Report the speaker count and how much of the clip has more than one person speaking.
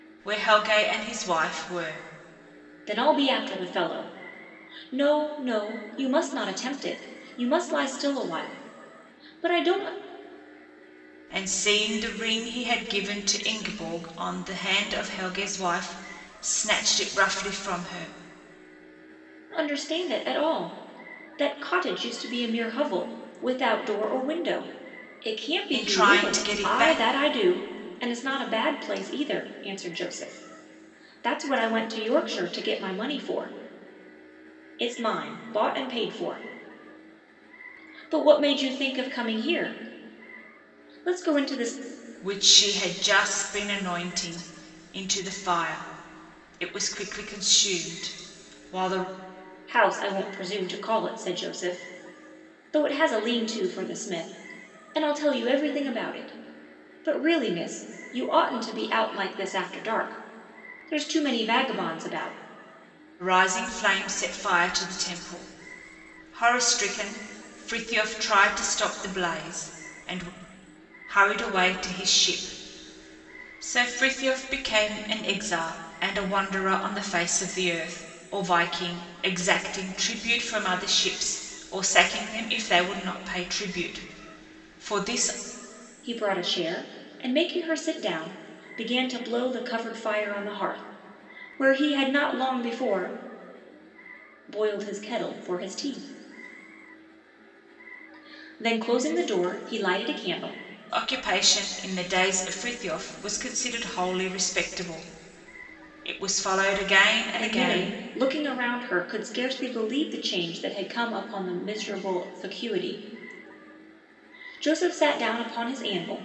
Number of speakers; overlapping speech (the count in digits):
2, about 2%